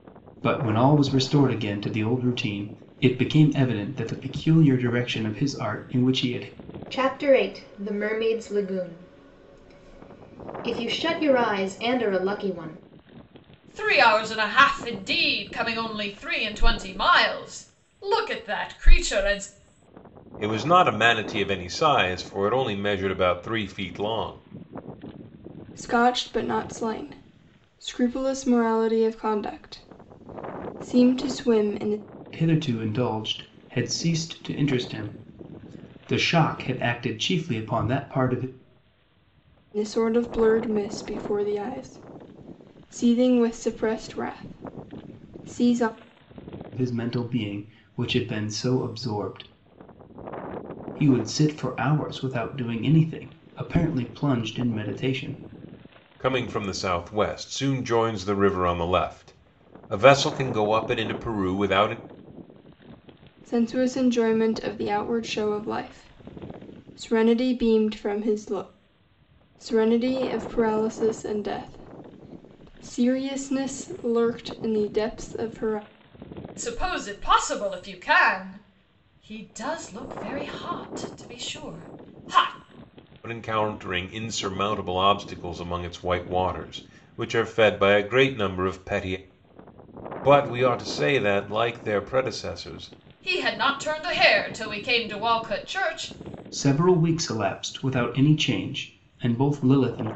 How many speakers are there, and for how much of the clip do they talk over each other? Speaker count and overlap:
five, no overlap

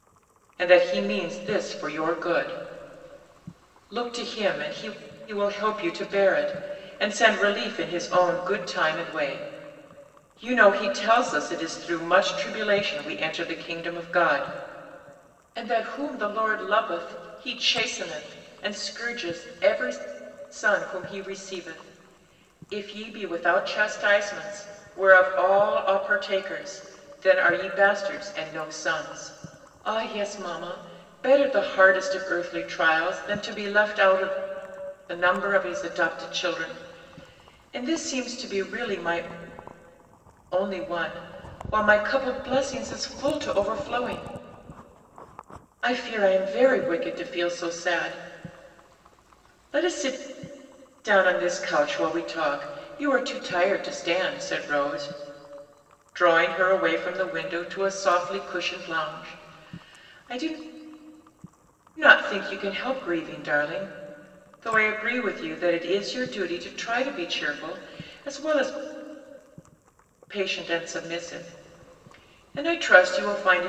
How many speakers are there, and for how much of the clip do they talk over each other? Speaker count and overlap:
one, no overlap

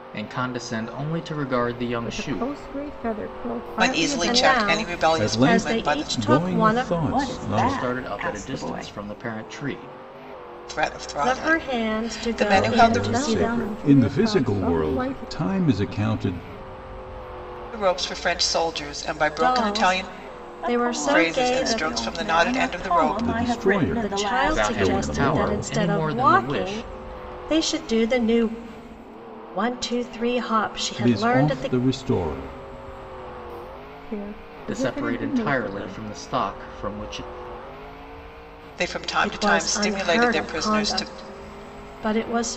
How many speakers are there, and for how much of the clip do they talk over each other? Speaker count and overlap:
six, about 49%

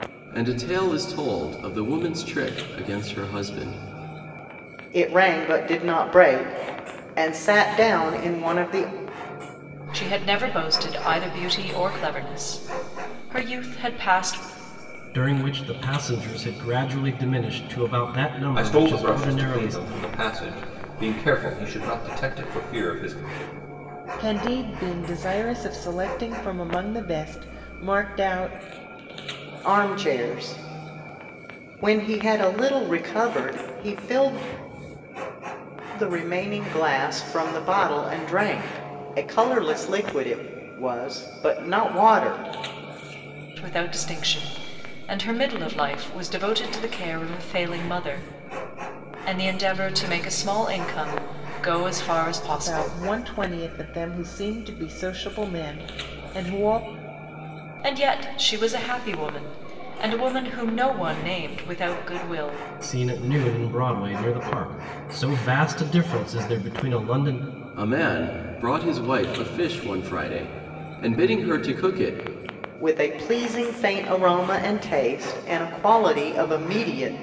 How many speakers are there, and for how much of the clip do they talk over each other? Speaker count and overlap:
six, about 2%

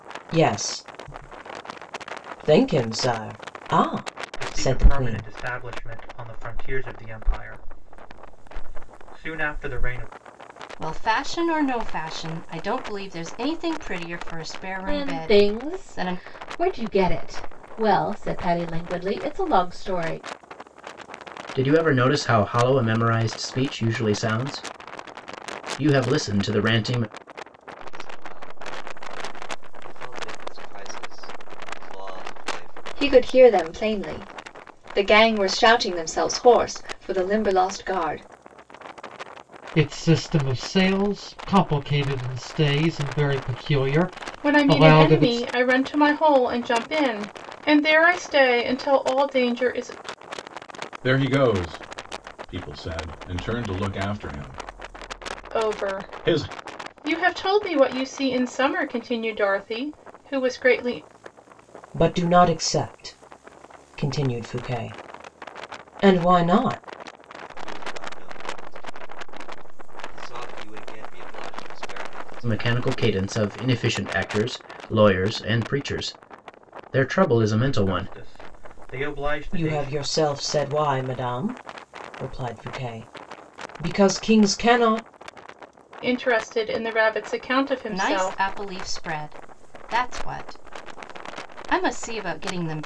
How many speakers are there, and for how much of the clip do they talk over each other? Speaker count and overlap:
ten, about 8%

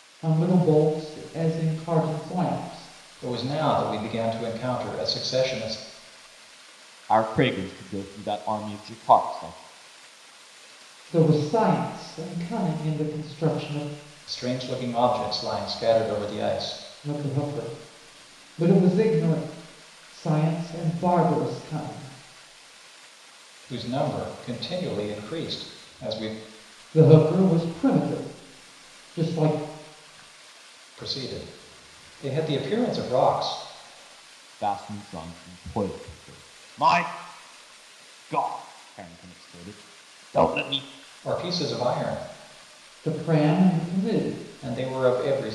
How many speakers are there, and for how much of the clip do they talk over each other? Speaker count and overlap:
three, no overlap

